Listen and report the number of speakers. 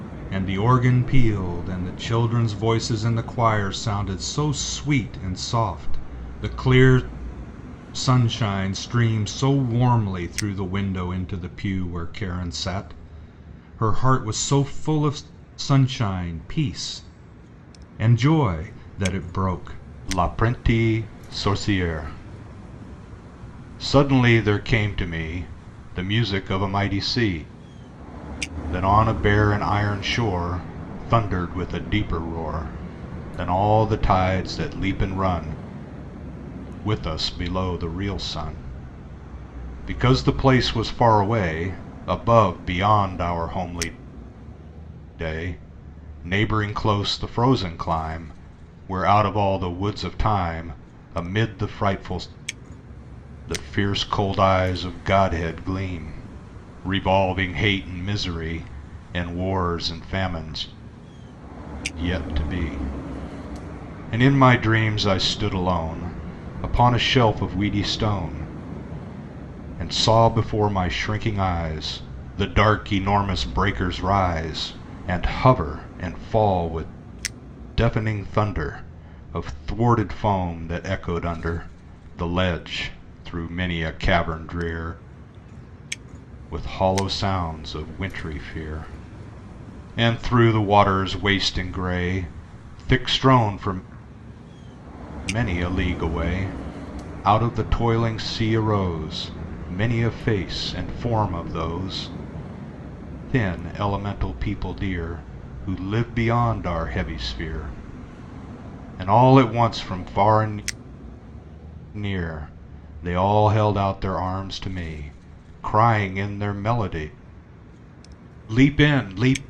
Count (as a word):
one